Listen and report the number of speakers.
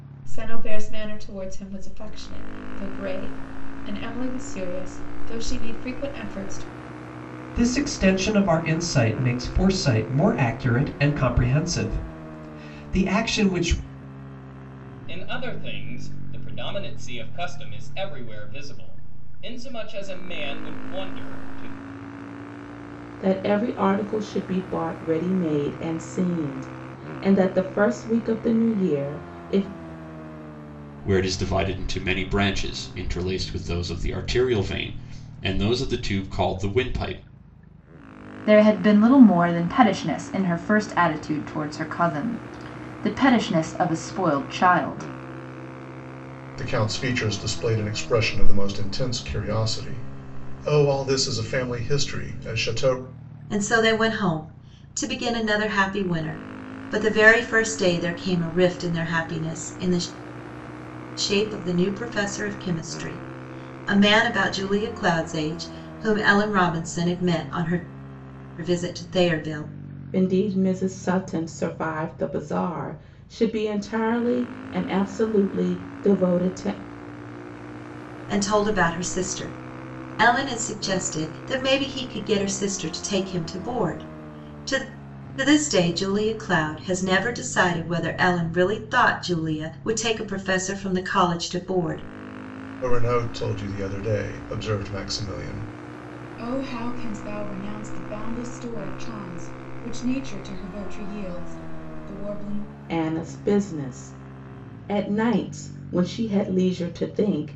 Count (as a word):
eight